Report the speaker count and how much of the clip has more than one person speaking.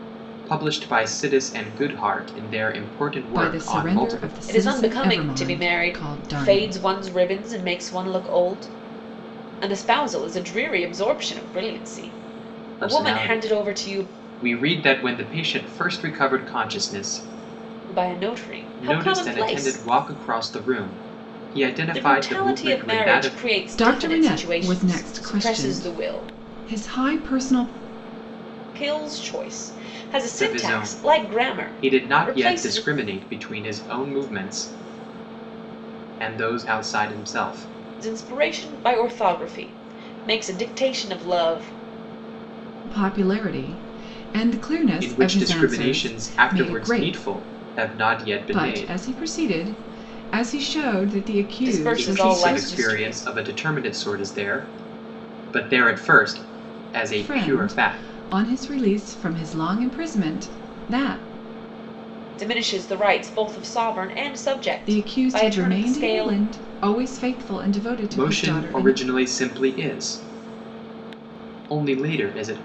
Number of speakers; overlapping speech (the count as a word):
three, about 28%